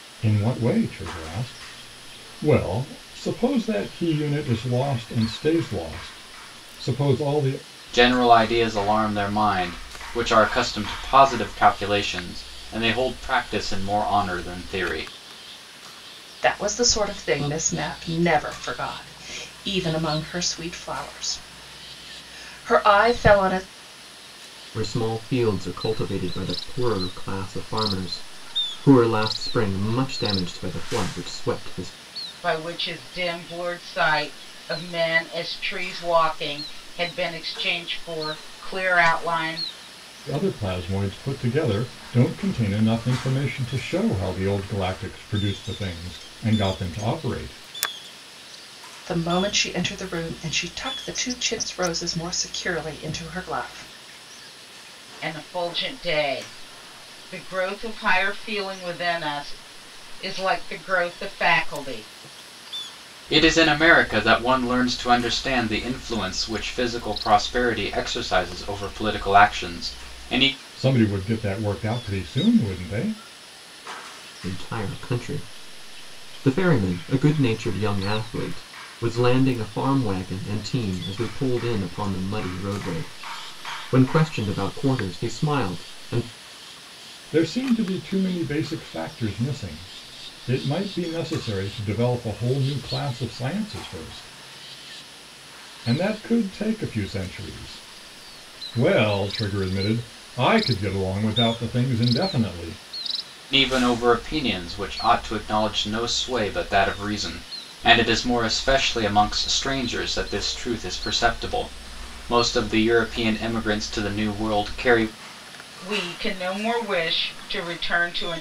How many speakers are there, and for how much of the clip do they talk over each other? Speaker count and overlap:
5, no overlap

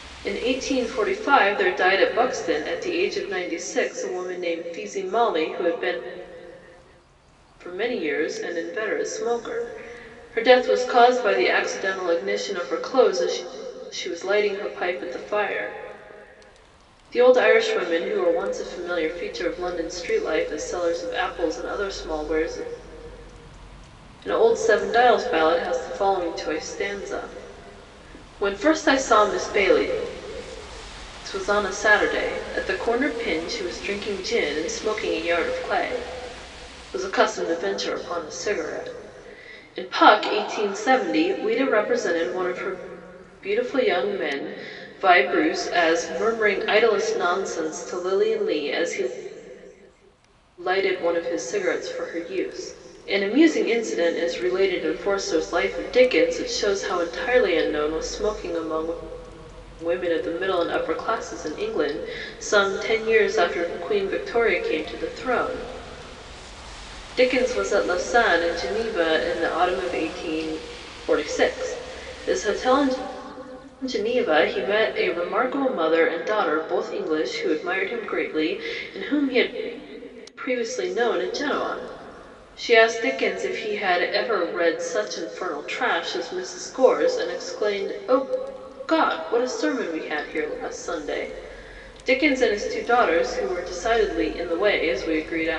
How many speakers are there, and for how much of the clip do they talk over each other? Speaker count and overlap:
1, no overlap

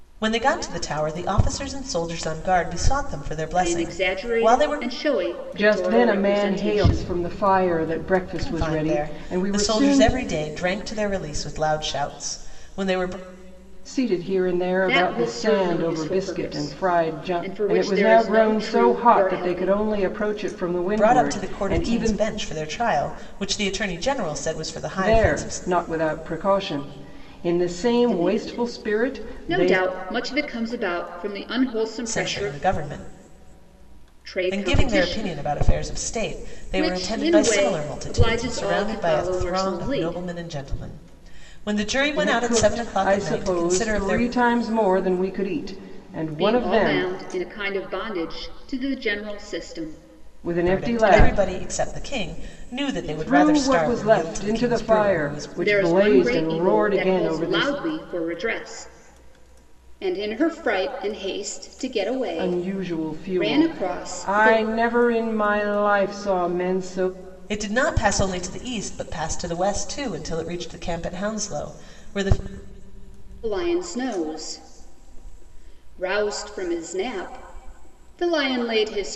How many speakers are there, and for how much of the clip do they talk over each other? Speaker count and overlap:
3, about 37%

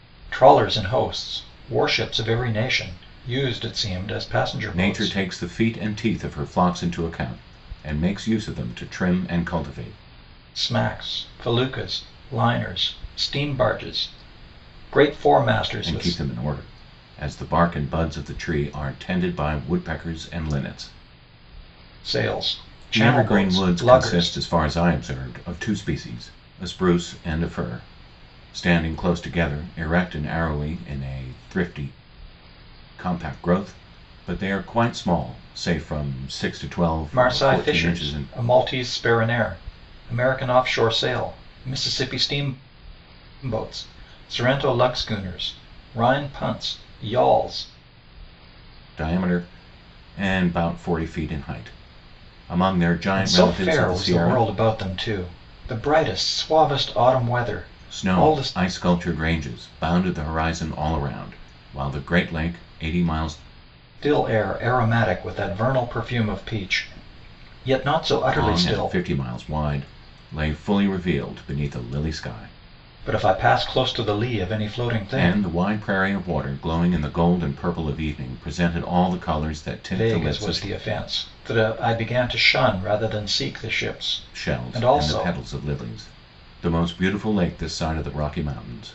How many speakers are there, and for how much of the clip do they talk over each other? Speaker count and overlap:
2, about 9%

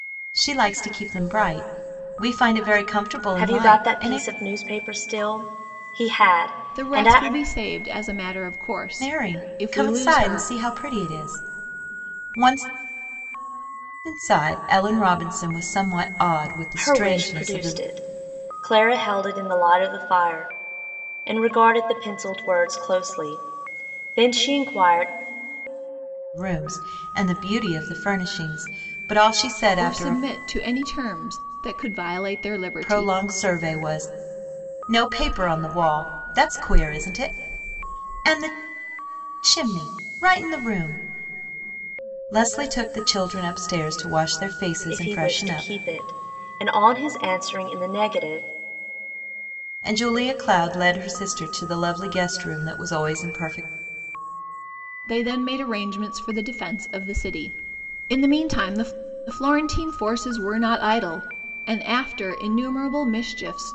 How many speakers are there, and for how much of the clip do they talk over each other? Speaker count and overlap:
3, about 9%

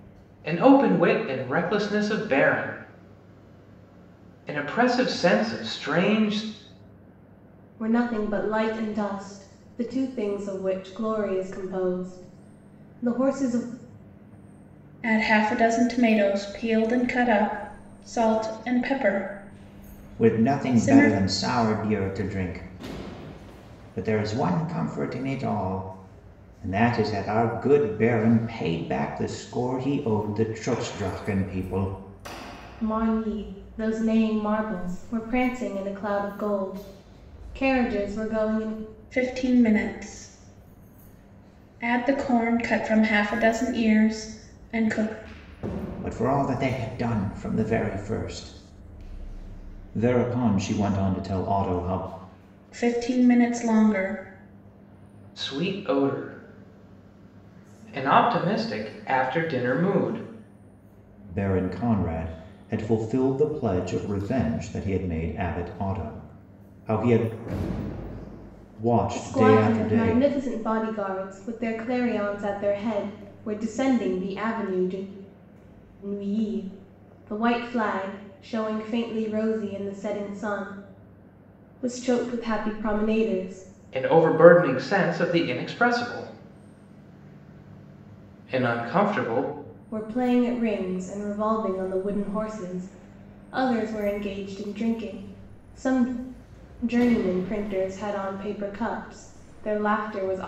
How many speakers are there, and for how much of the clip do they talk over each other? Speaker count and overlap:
4, about 2%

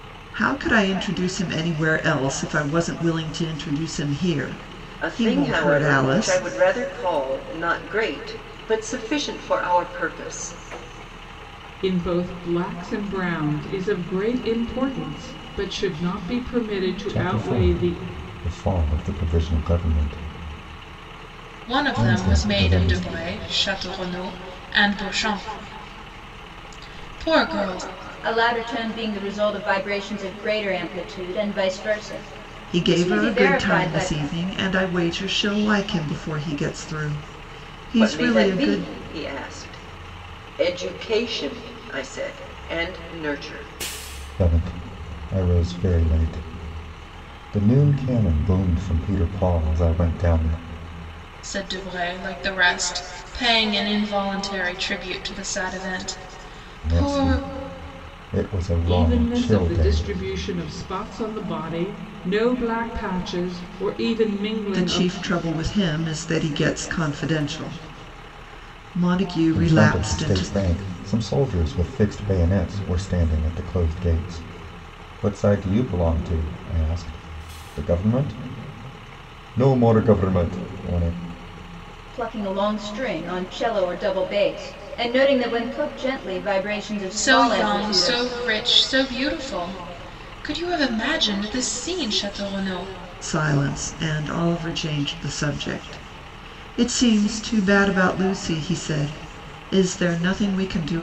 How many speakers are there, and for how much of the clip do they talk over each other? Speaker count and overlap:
6, about 10%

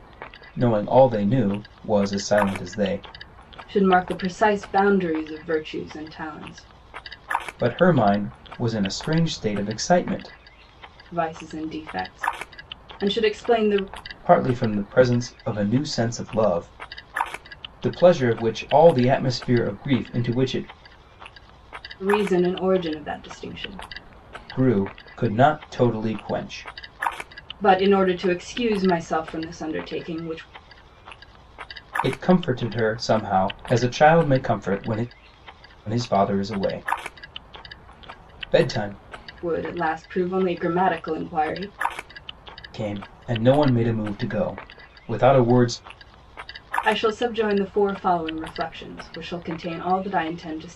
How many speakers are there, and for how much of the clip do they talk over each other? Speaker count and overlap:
2, no overlap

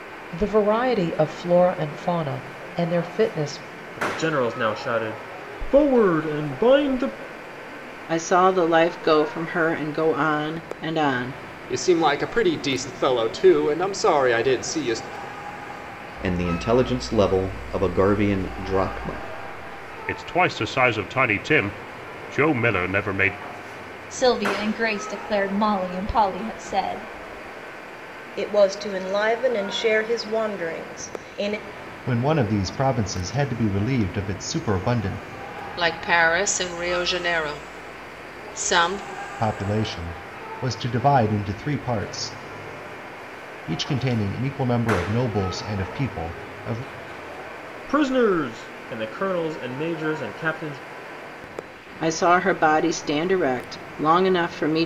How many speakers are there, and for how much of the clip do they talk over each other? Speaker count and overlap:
10, no overlap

